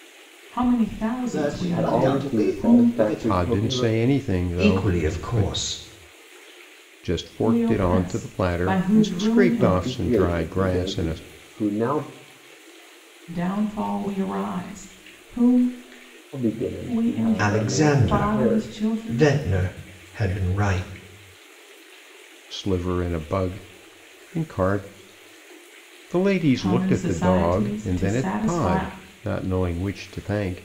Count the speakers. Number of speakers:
5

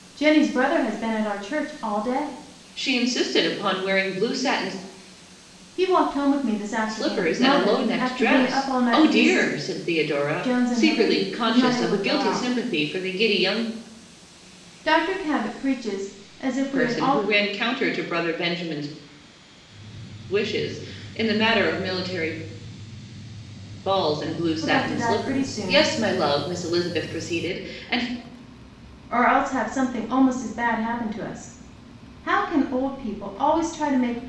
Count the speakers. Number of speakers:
2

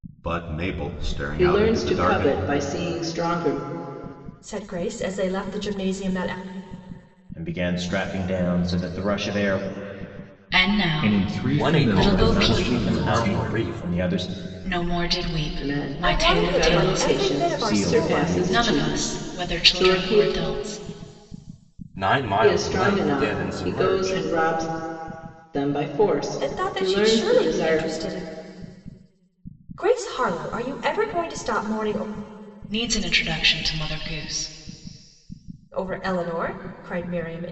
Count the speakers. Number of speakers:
7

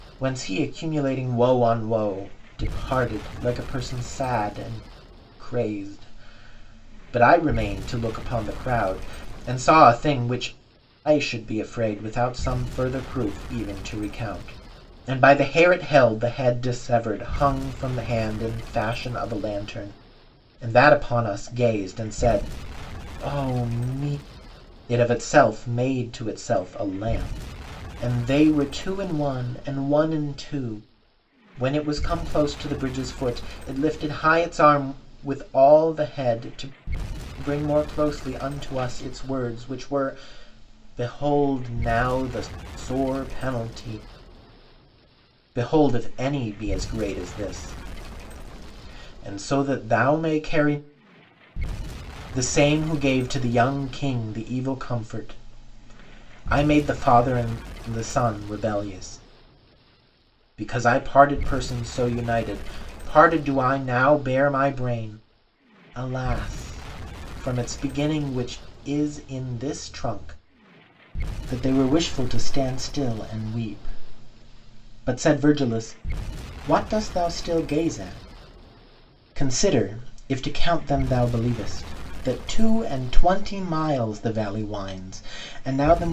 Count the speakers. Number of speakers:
1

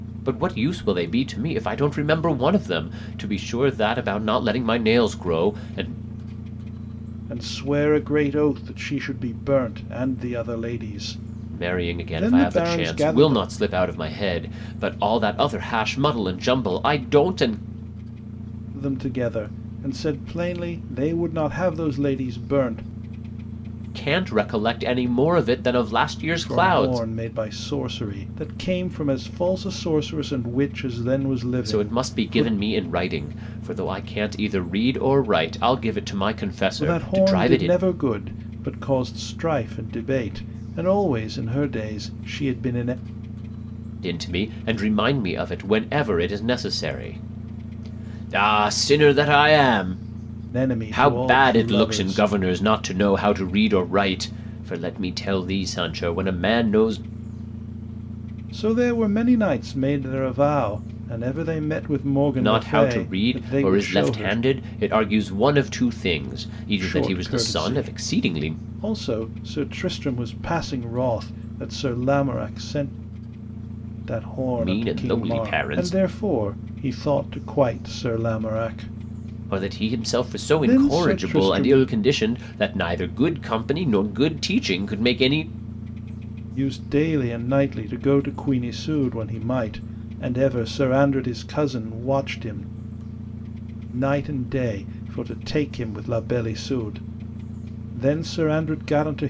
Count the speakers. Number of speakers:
2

